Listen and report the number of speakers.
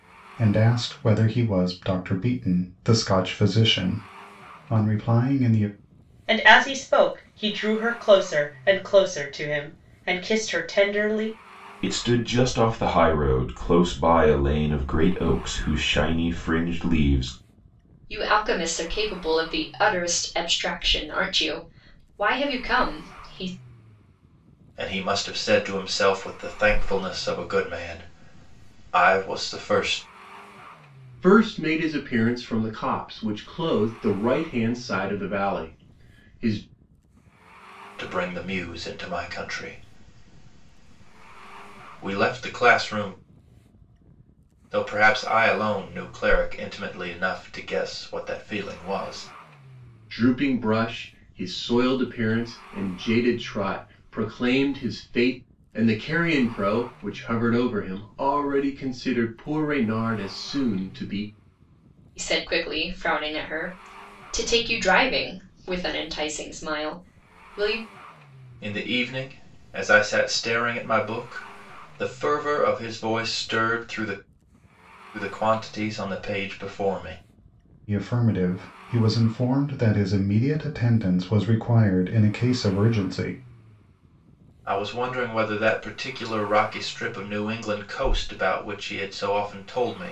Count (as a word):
six